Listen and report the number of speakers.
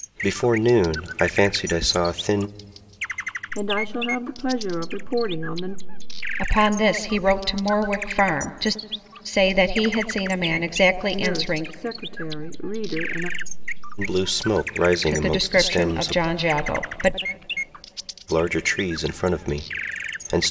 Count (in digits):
3